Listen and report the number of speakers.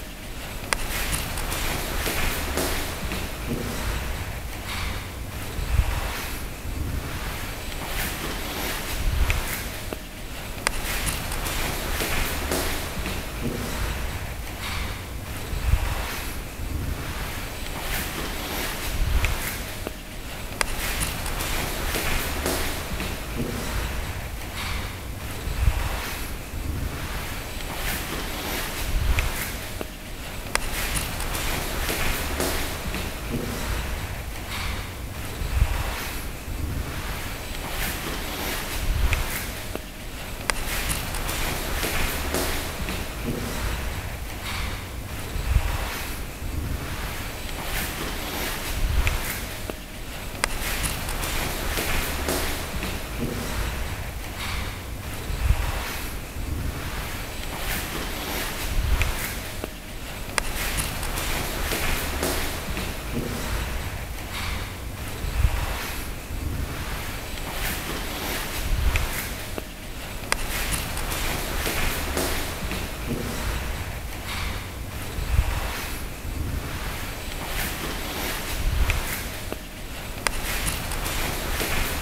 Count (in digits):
0